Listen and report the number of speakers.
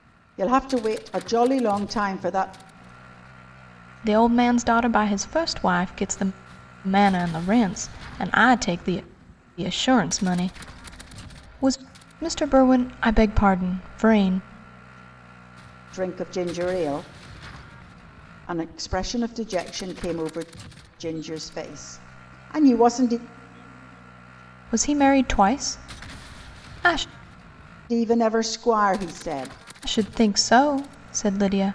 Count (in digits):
2